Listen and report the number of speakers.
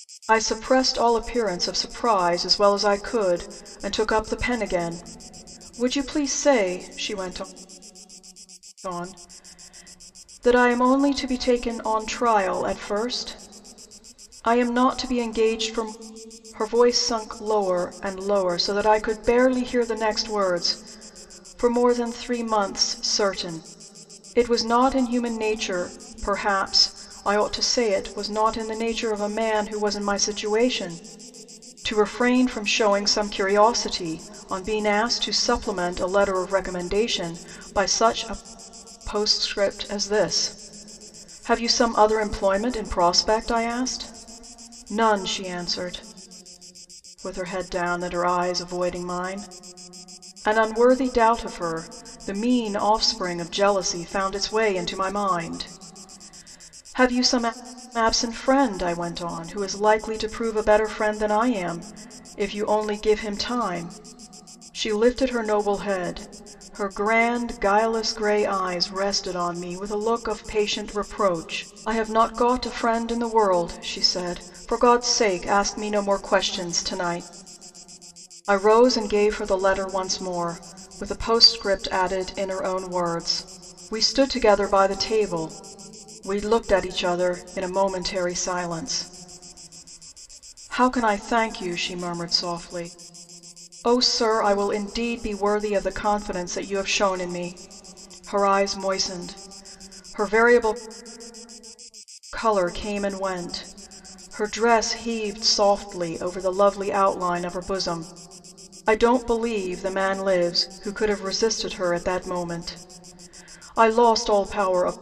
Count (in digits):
1